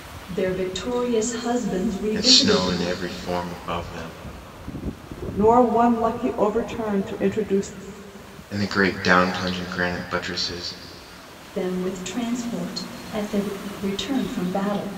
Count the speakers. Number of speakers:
3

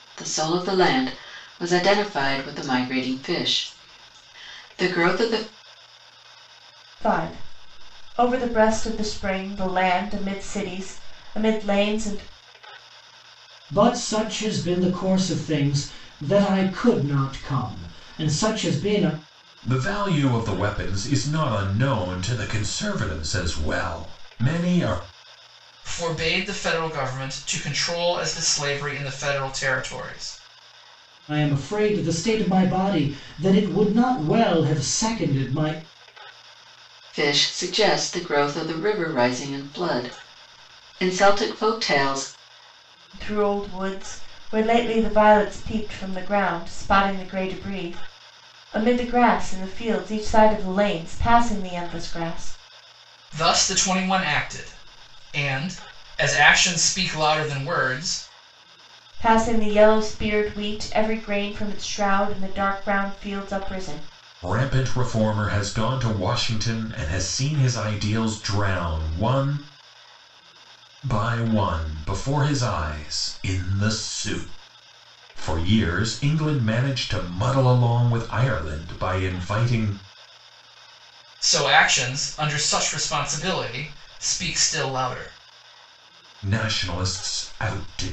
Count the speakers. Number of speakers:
5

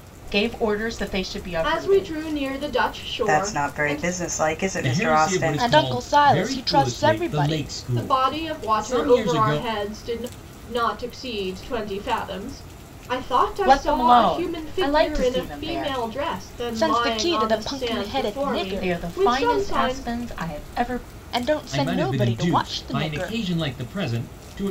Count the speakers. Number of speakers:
5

